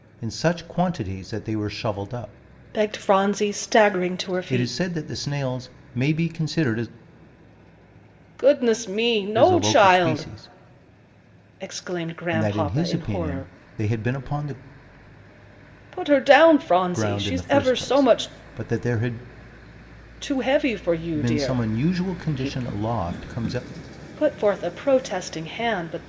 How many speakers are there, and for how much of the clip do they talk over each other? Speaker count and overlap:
two, about 21%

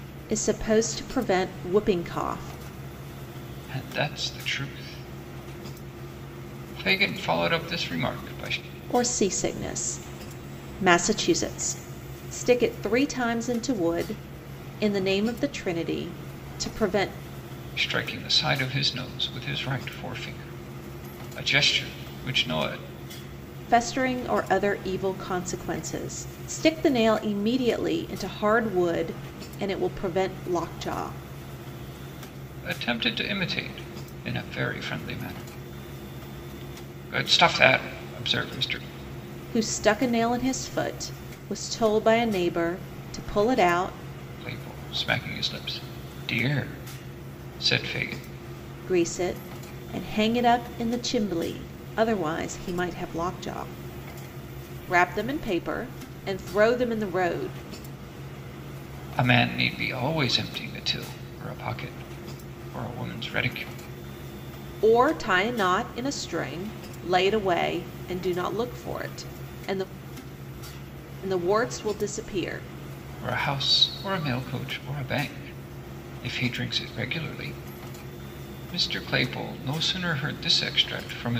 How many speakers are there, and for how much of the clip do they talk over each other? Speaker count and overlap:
two, no overlap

